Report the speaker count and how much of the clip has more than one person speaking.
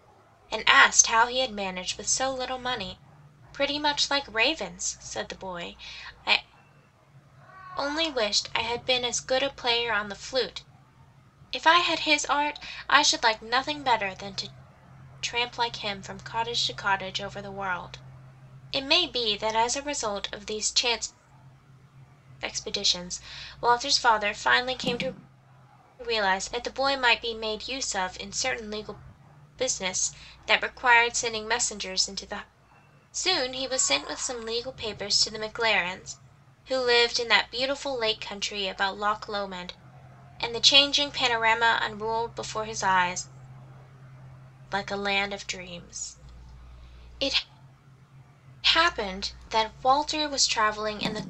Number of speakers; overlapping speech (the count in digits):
1, no overlap